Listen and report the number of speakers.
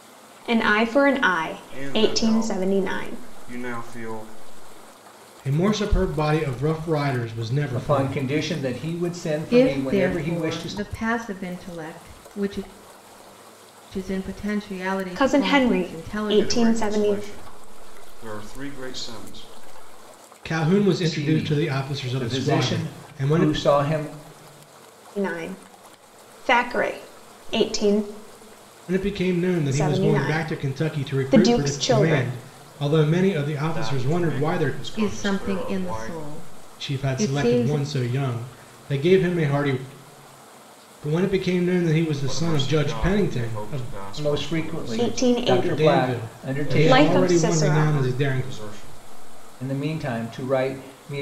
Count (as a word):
five